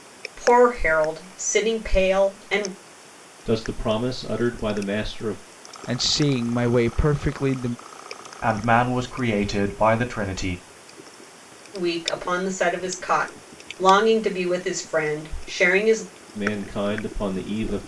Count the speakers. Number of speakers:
four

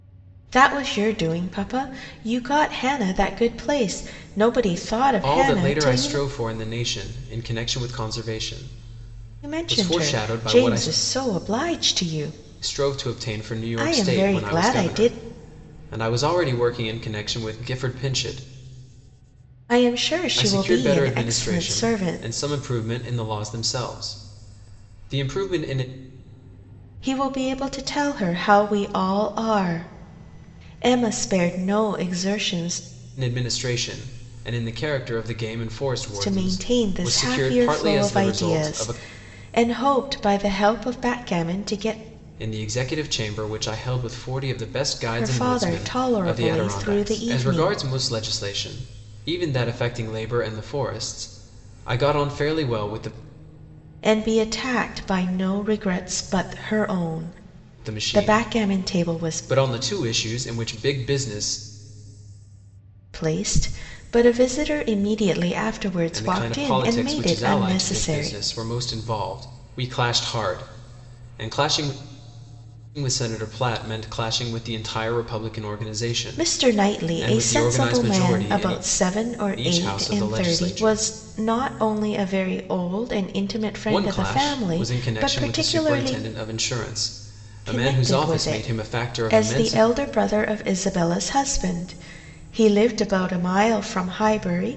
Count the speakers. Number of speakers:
two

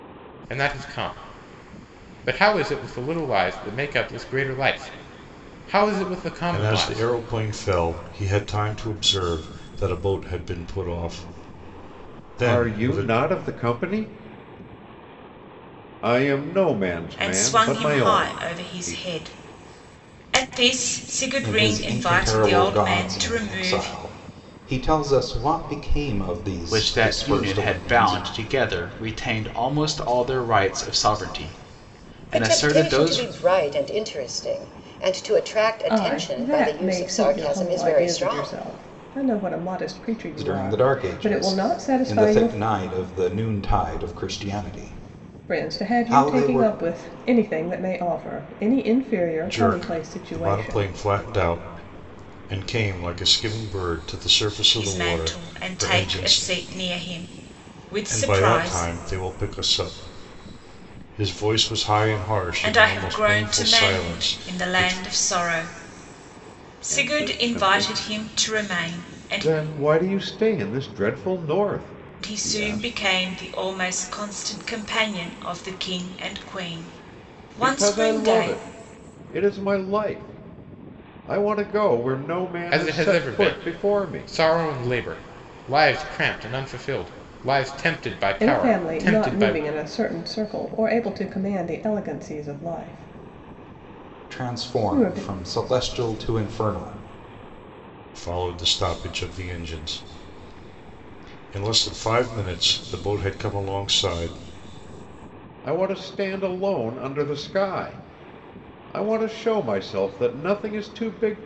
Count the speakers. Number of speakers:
eight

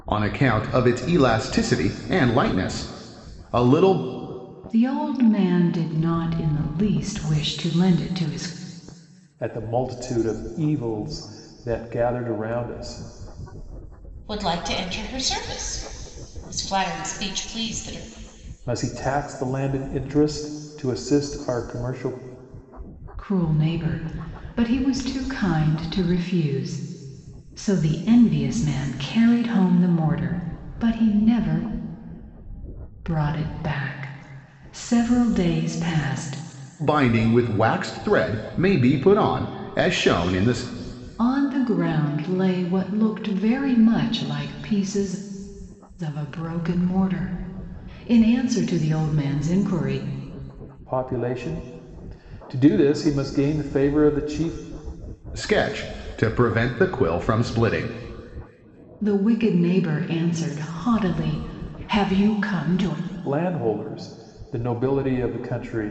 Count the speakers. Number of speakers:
four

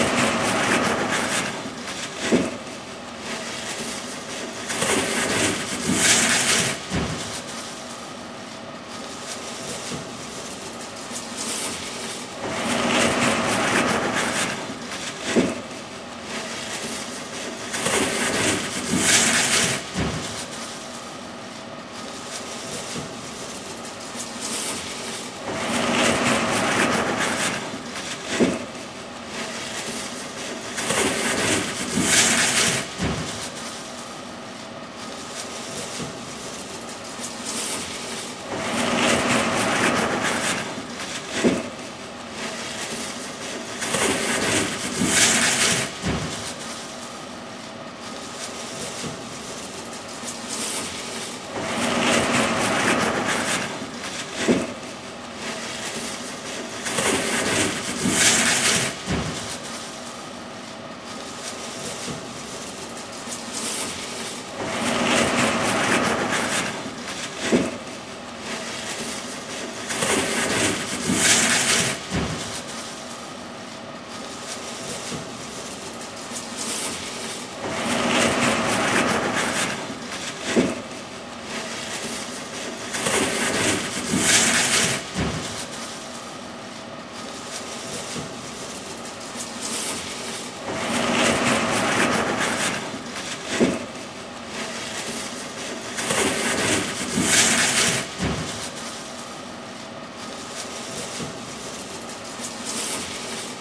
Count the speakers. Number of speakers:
zero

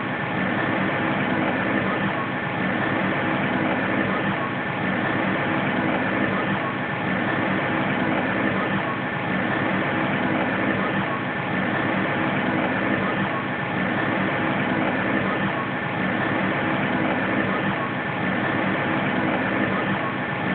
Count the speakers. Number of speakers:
zero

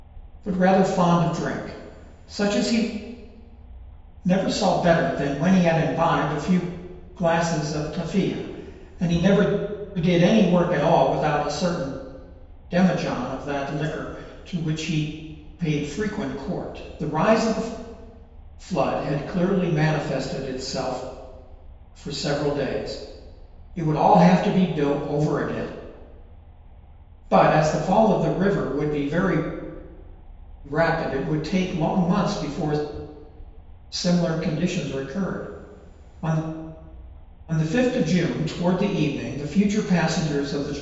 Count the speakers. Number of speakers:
one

